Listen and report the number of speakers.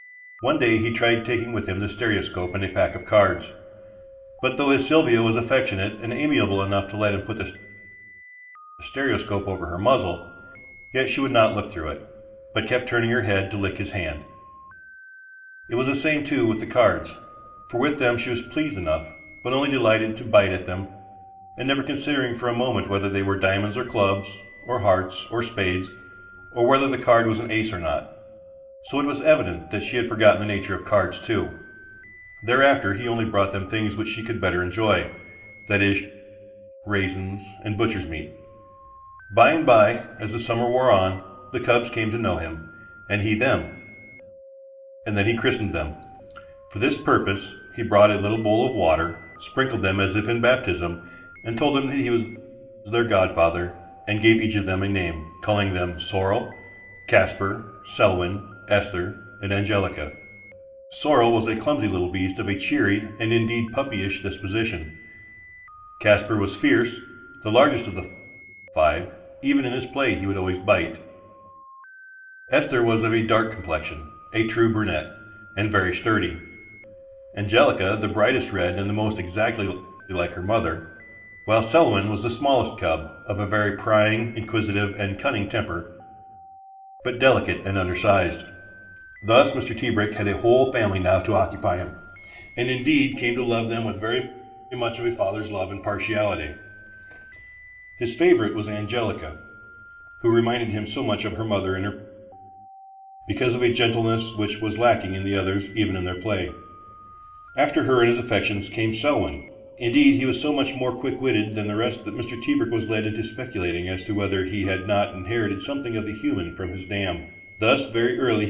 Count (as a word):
one